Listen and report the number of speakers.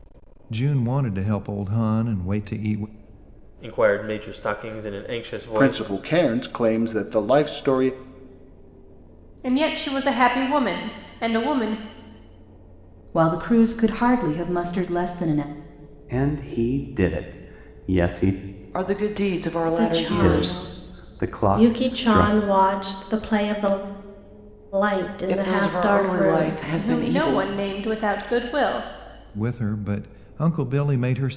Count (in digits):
8